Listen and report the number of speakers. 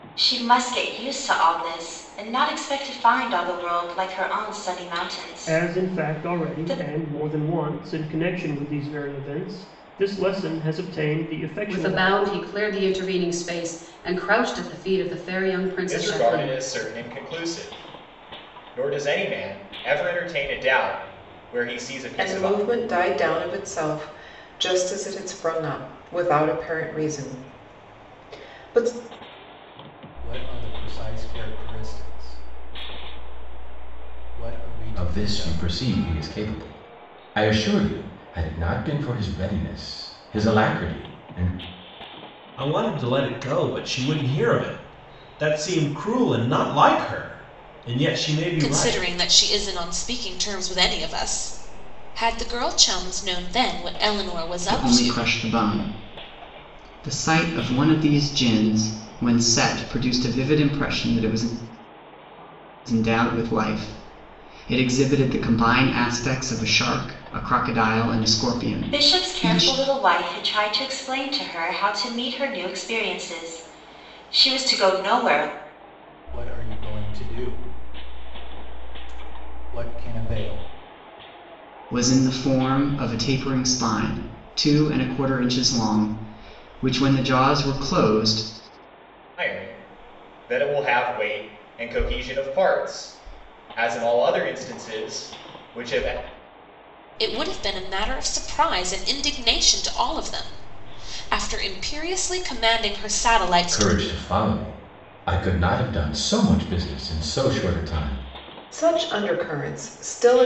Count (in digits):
10